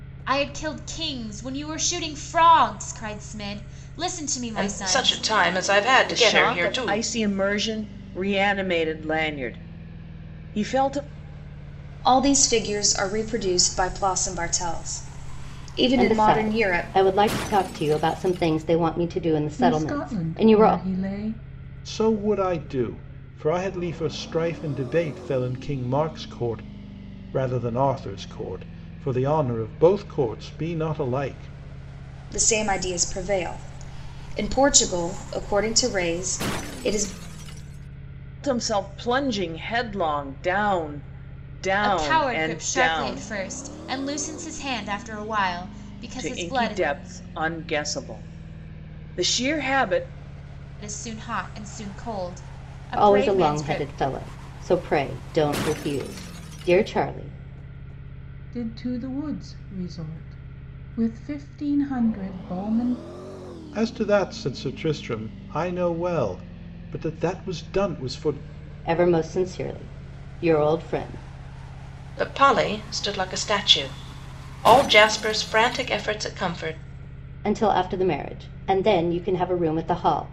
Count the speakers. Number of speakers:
seven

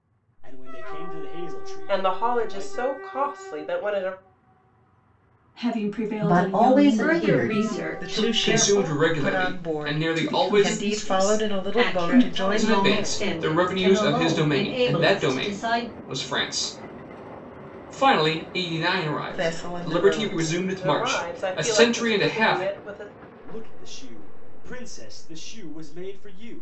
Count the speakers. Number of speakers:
seven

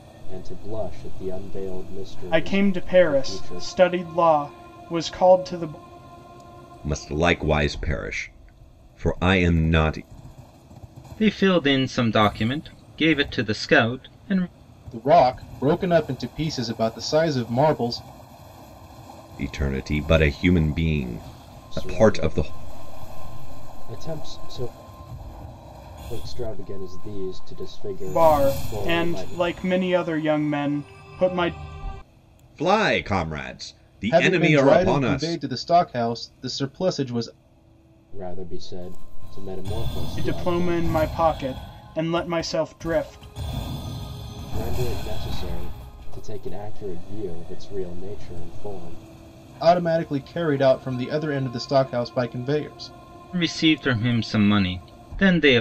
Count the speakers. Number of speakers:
five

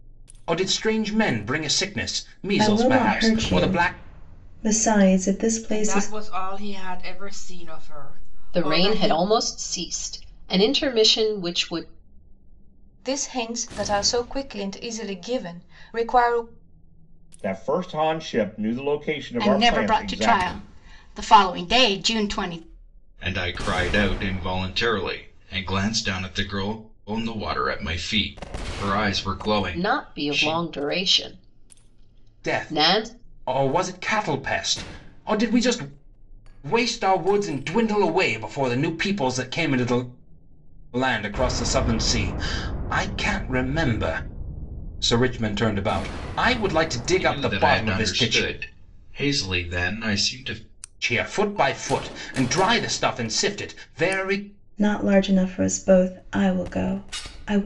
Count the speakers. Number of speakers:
eight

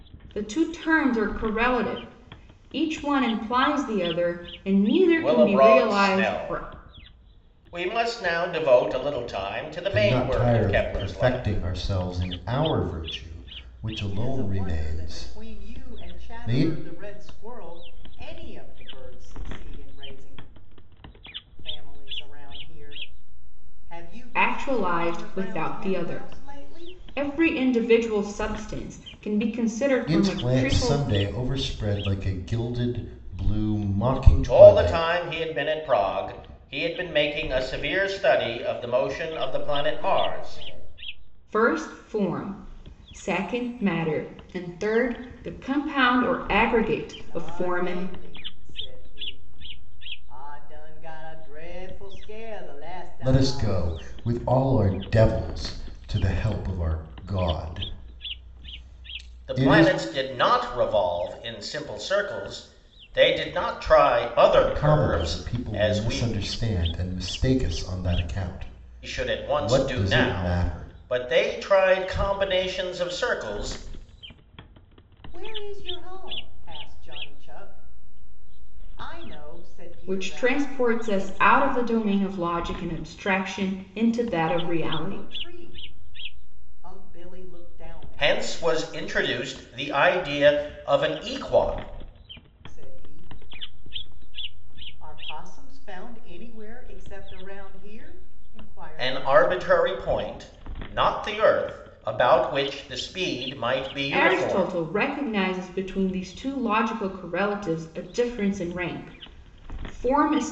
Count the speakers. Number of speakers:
four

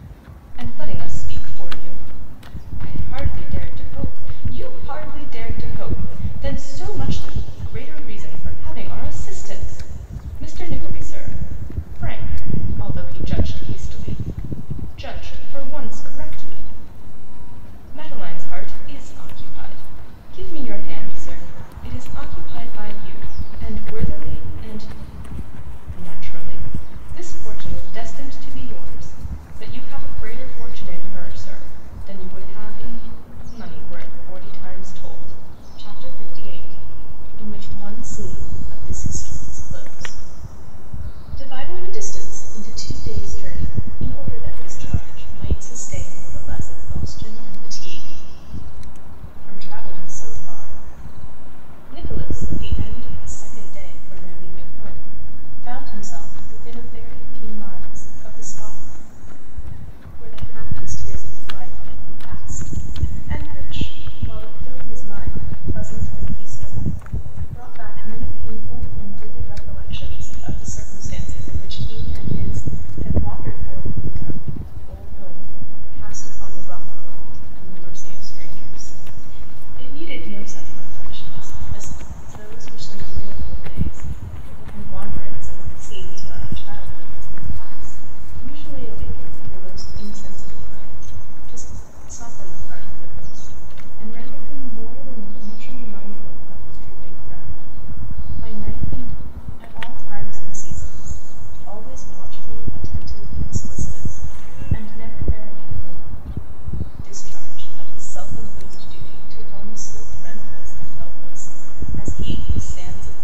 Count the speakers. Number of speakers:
one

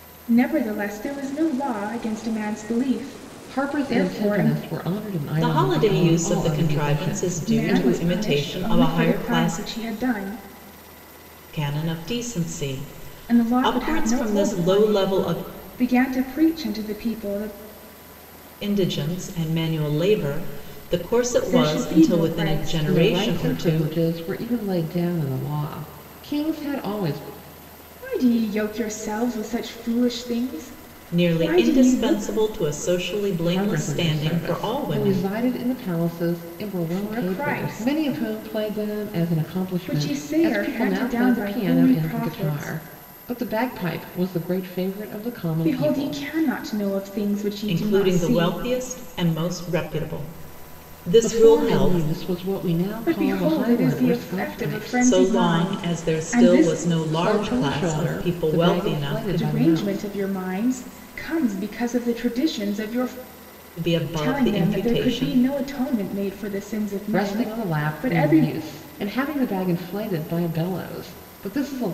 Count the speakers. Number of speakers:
three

